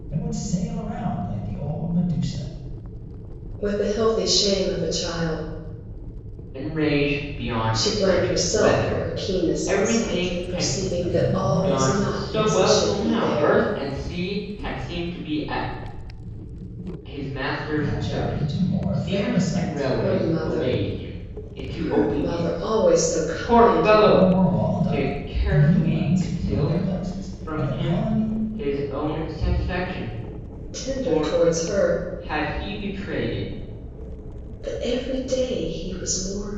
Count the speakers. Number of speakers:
three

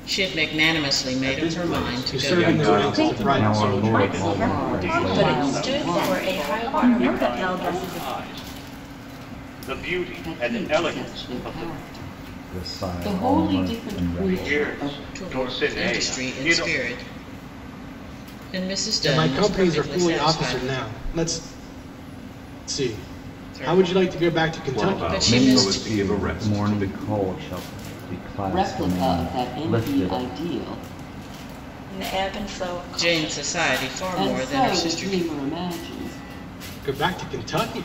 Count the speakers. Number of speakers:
nine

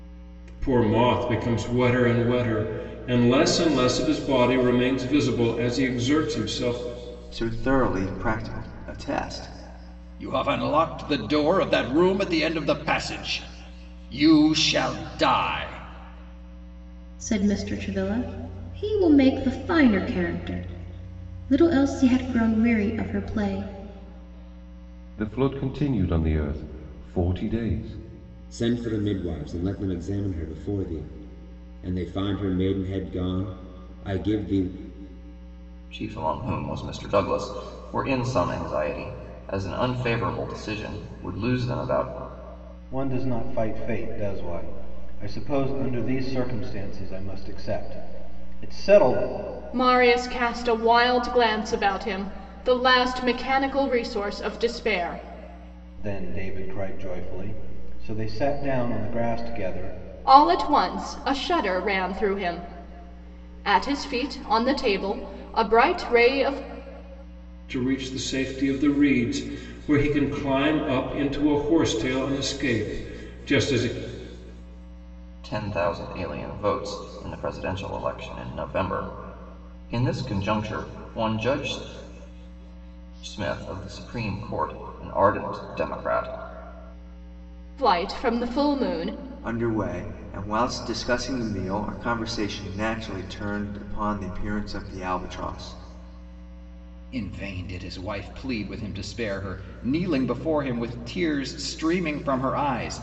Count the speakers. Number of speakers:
nine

